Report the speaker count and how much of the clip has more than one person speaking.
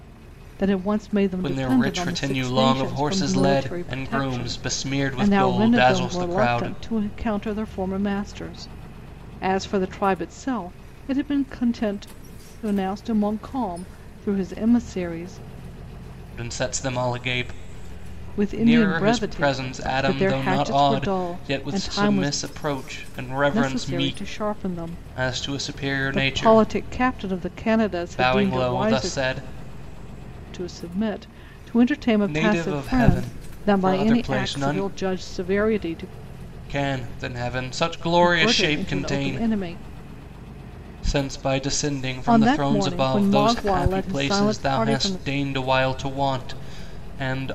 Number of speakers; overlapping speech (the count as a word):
two, about 40%